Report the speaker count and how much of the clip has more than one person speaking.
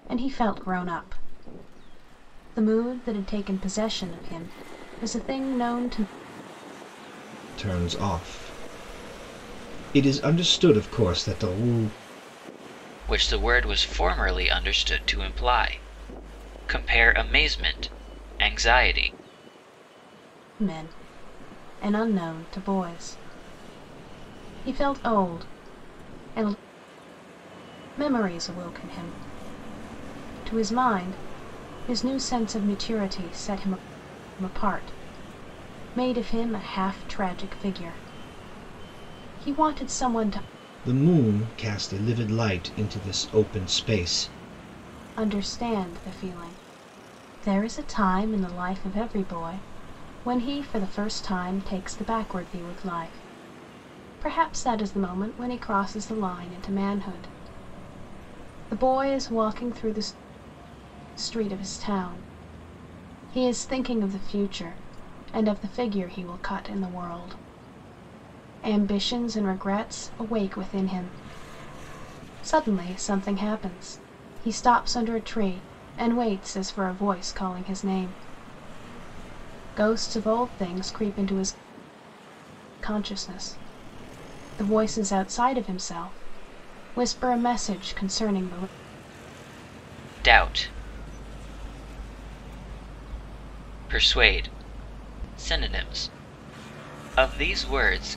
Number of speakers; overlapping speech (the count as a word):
three, no overlap